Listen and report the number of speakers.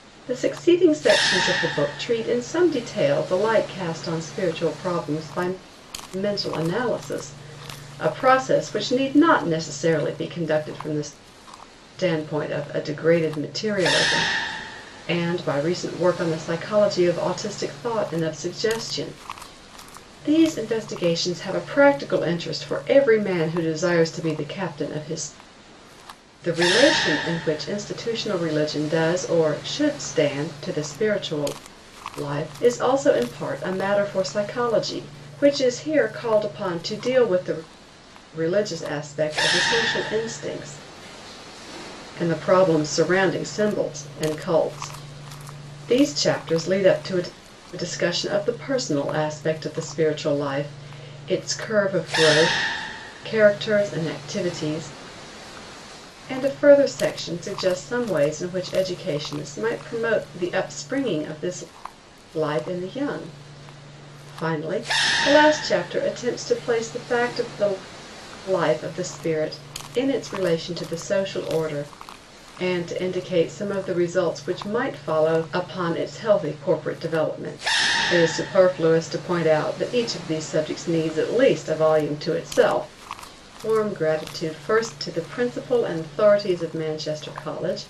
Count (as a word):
one